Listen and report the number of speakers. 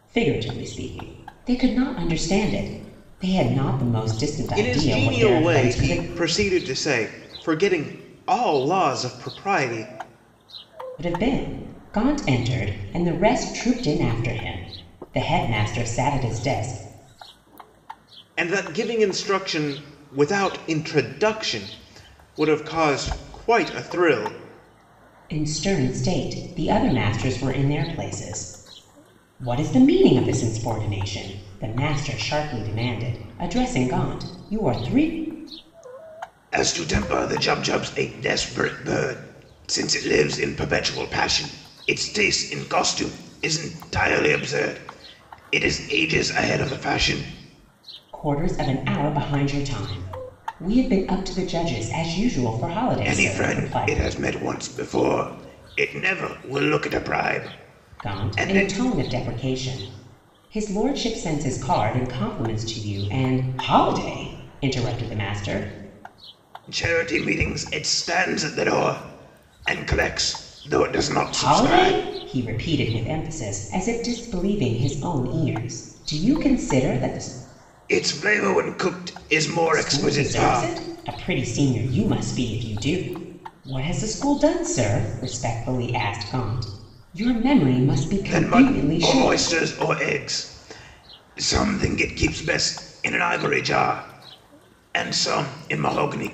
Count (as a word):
two